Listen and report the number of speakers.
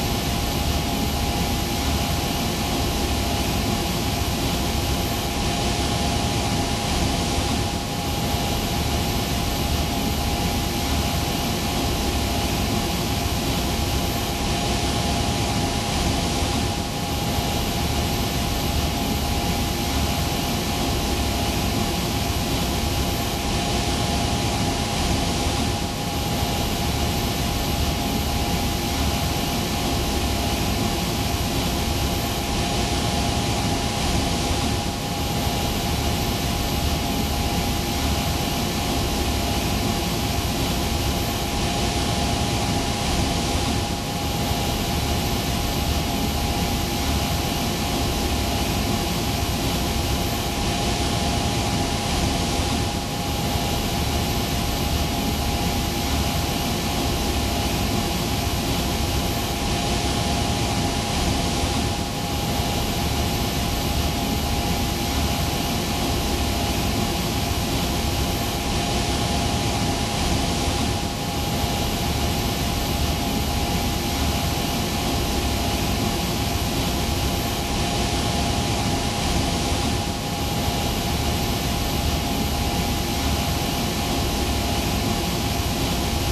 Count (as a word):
zero